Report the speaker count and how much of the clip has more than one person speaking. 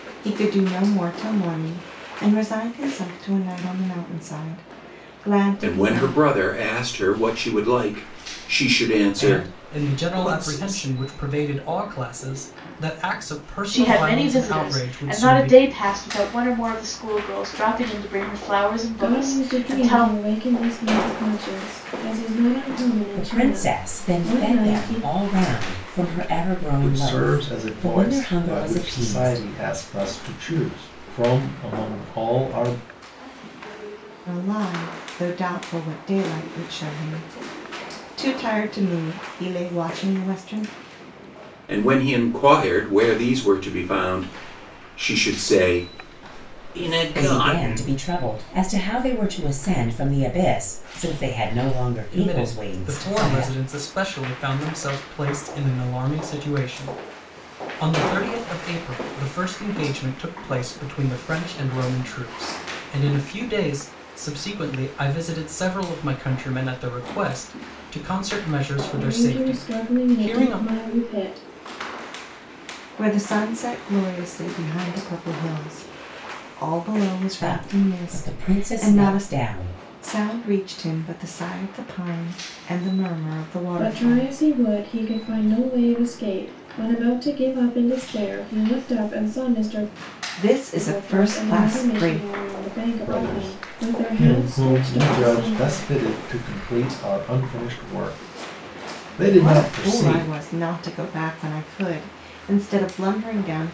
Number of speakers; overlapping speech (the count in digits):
7, about 21%